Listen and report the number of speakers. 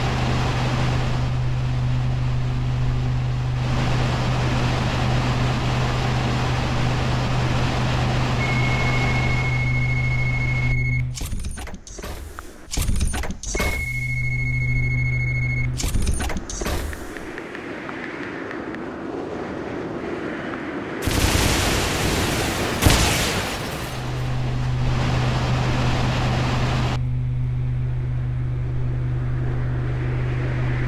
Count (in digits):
0